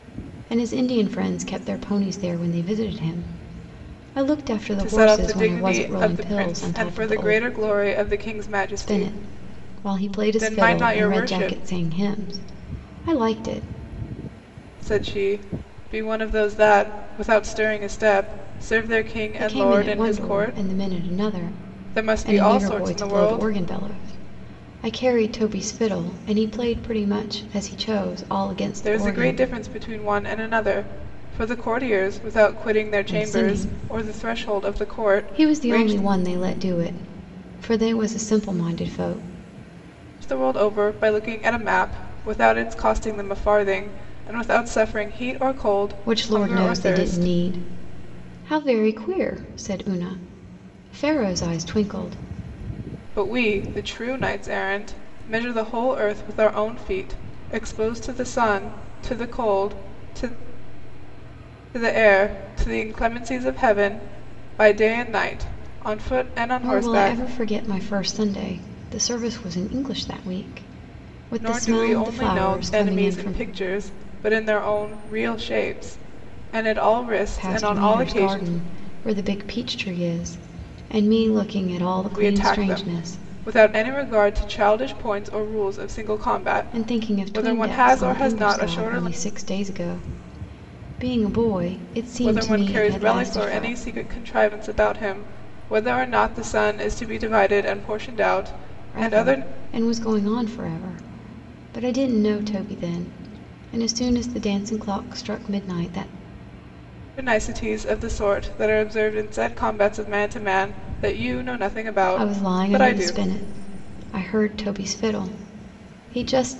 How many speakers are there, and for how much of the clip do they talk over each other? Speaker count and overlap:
2, about 21%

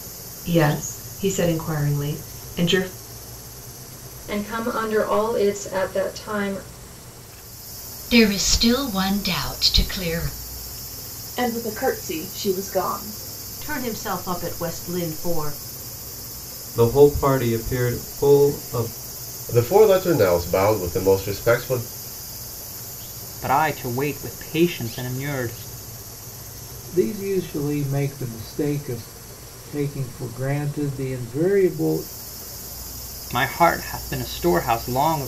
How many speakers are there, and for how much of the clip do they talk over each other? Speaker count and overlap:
9, no overlap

